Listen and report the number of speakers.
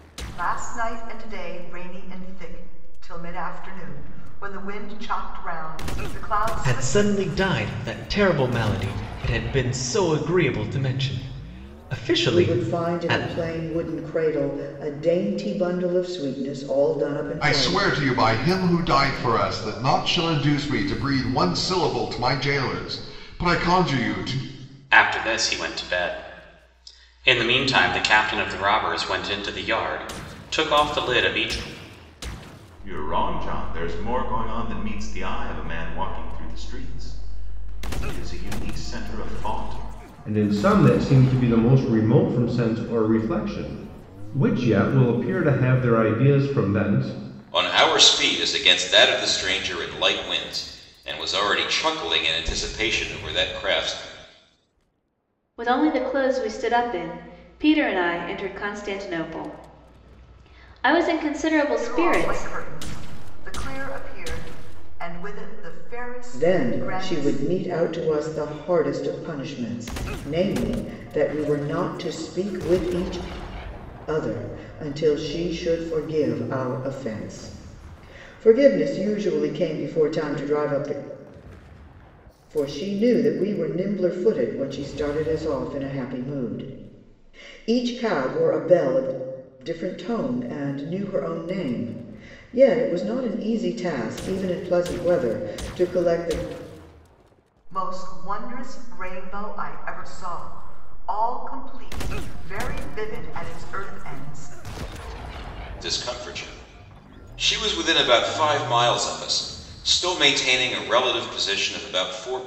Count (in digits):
9